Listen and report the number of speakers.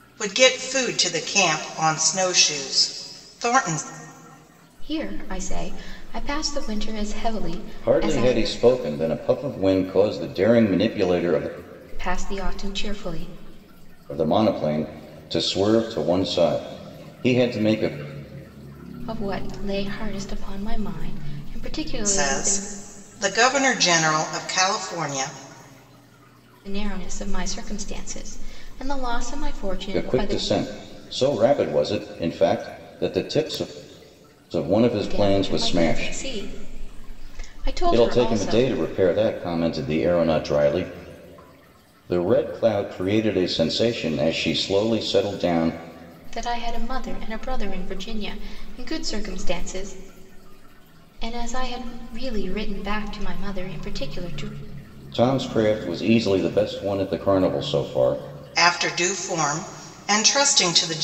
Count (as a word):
three